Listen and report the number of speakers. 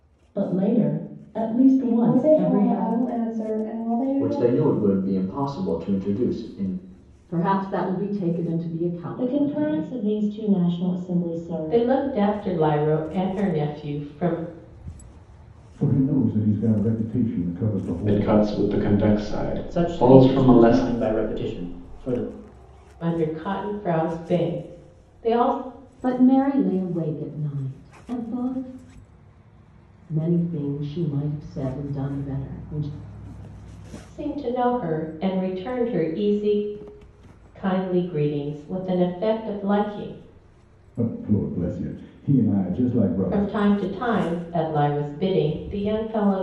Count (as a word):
nine